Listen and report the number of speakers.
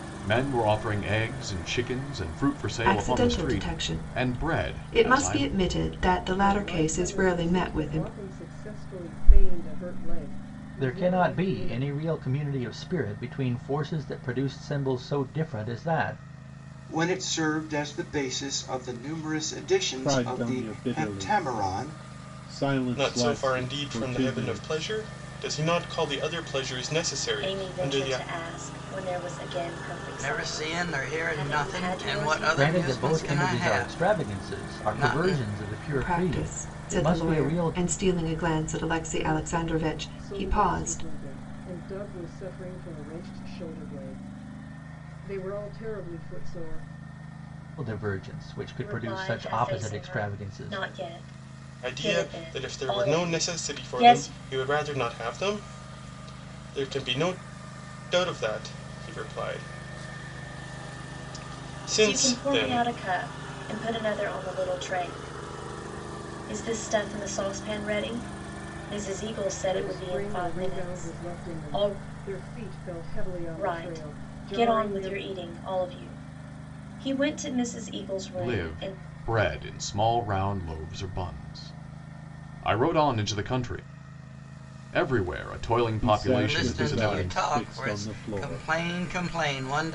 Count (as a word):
nine